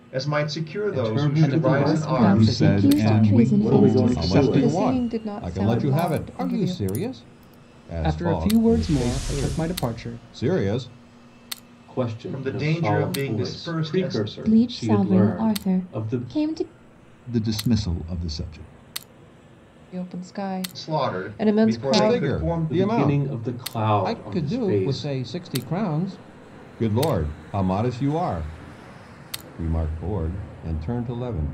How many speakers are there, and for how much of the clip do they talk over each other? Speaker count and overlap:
8, about 52%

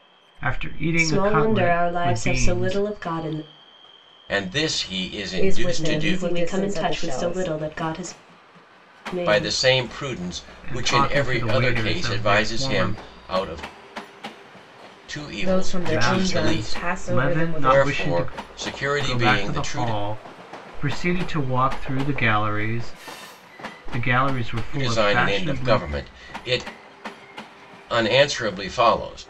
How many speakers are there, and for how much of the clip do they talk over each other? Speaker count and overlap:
4, about 40%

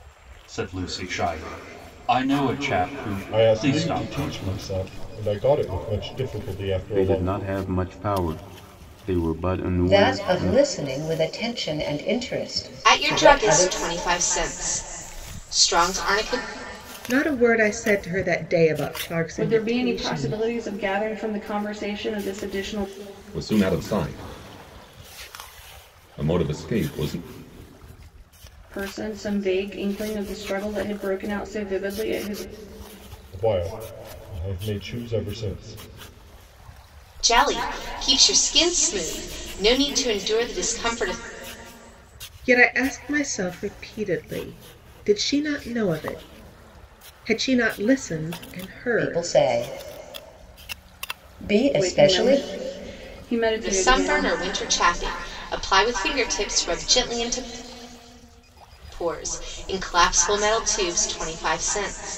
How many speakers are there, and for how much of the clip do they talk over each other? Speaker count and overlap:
8, about 10%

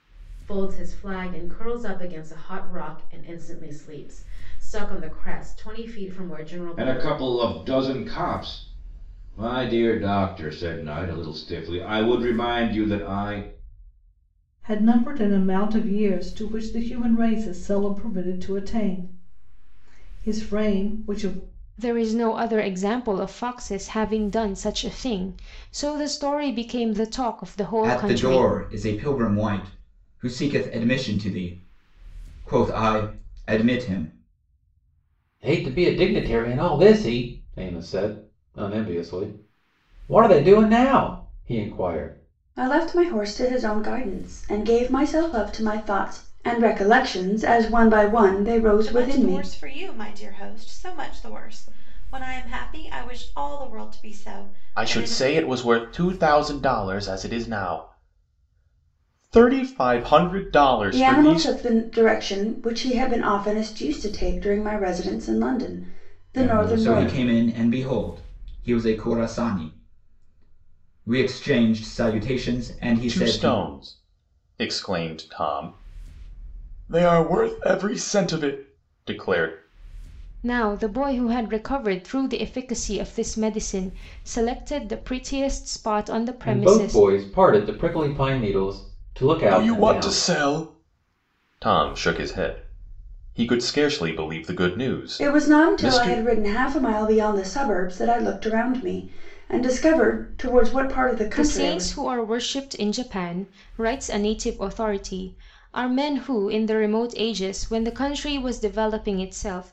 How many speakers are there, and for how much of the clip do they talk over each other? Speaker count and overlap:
9, about 7%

